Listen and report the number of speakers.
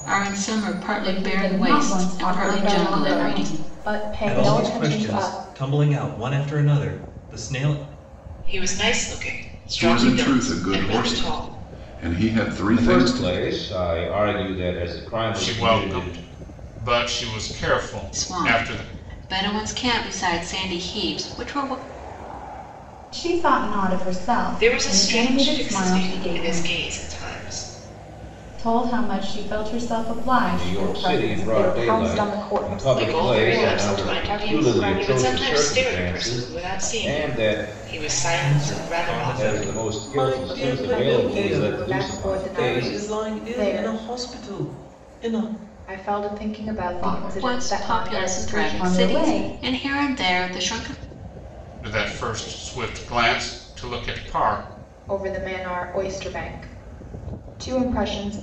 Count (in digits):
8